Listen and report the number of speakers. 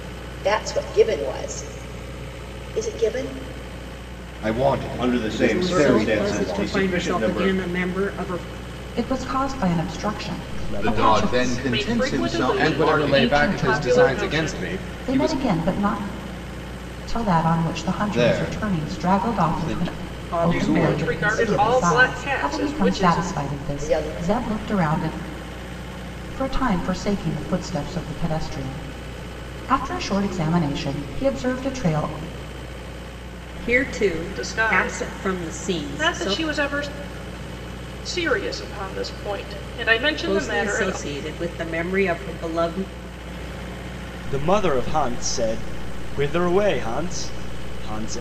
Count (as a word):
nine